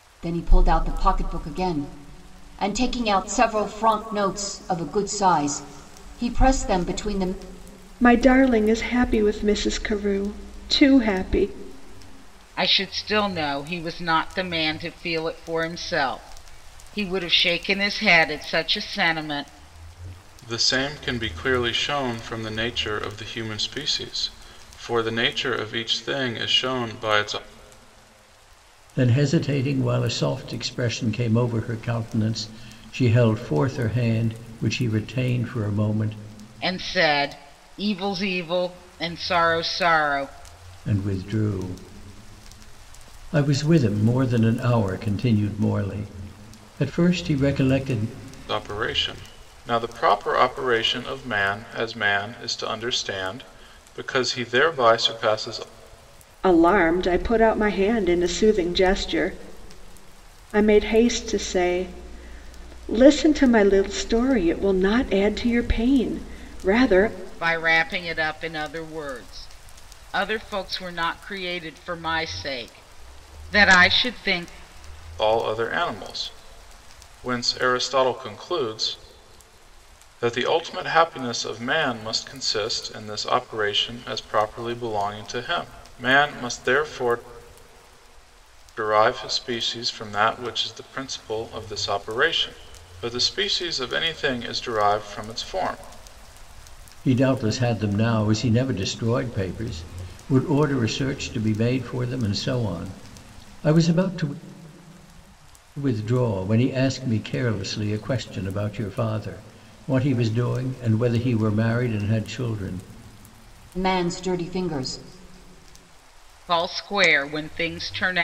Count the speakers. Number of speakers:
five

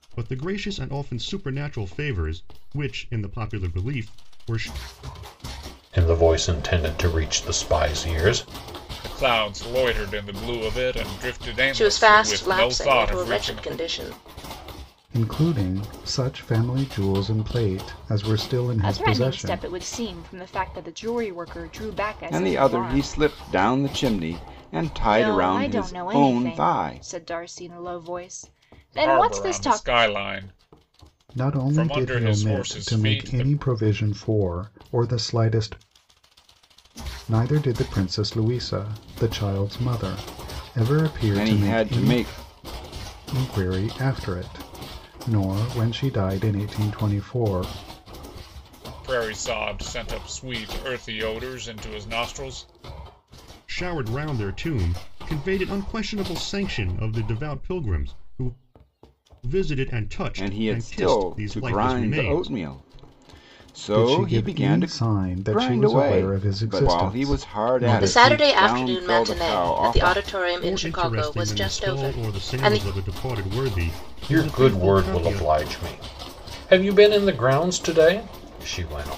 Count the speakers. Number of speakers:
seven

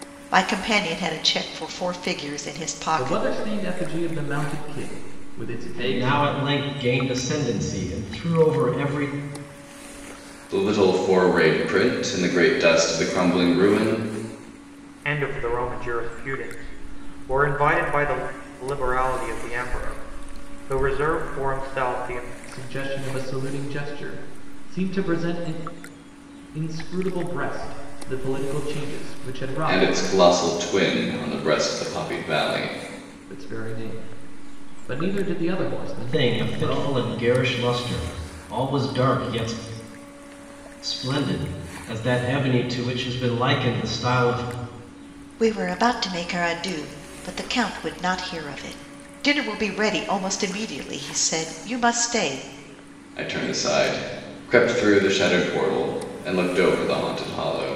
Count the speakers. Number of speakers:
five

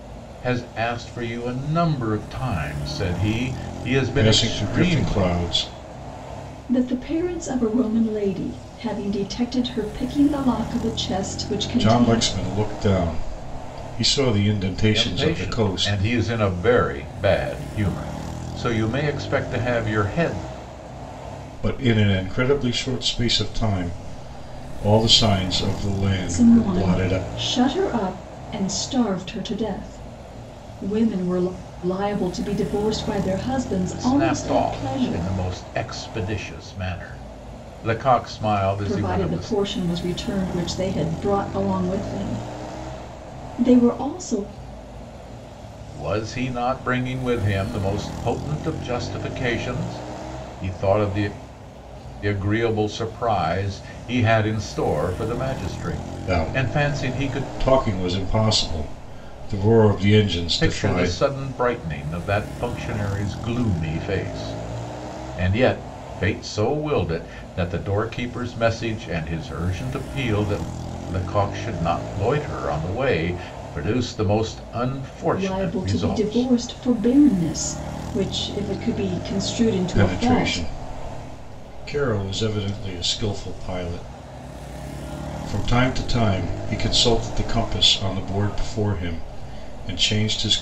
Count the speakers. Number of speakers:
three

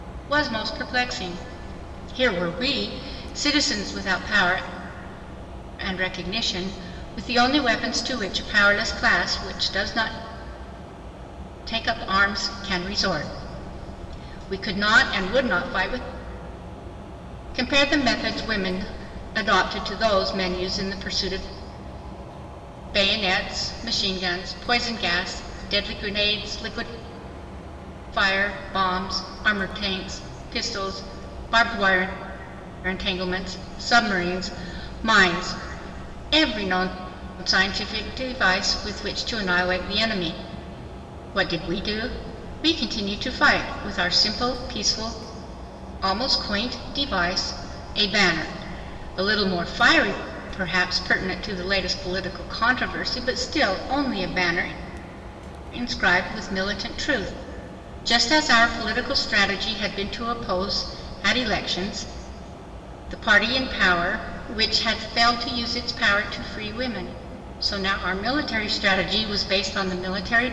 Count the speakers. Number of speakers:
one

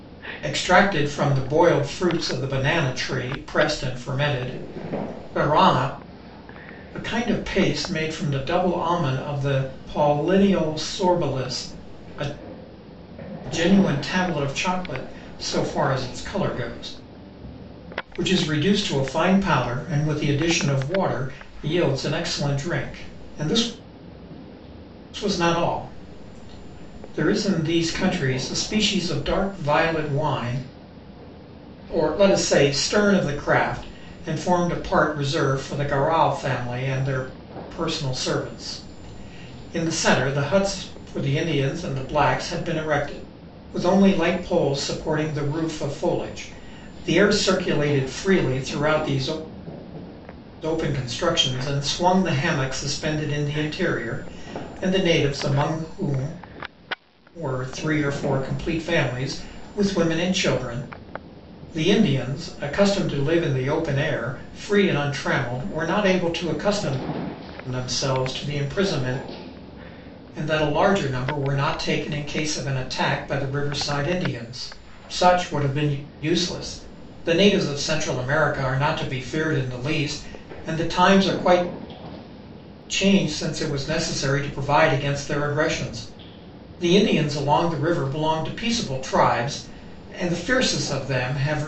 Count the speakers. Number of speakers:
one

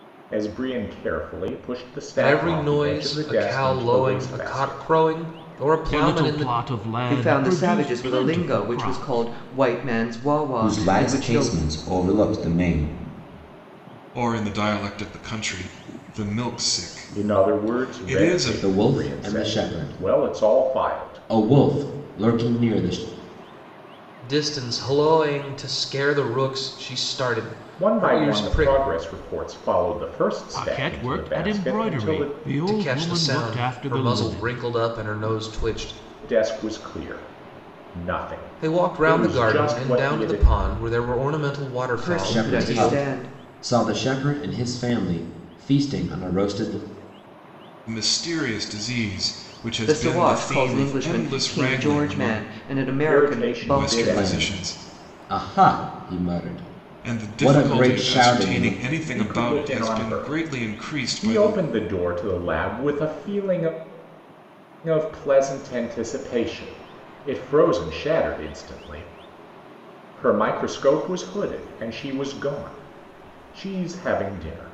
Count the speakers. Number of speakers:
six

